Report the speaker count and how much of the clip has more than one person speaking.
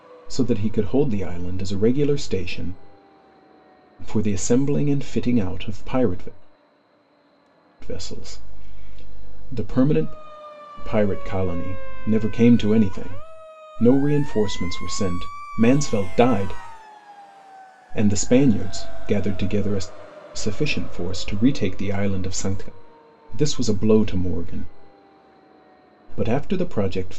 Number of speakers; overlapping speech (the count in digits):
1, no overlap